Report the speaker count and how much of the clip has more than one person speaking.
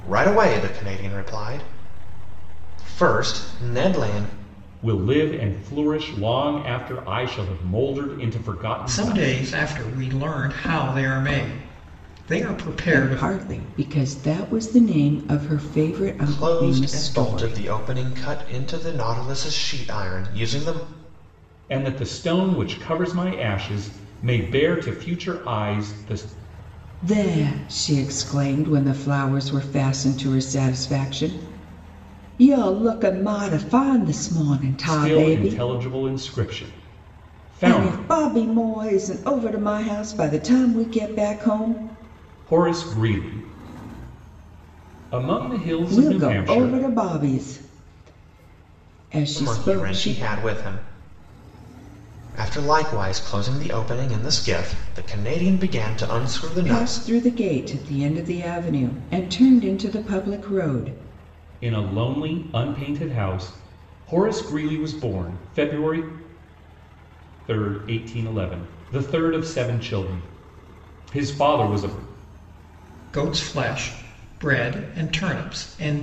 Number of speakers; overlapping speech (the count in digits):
4, about 8%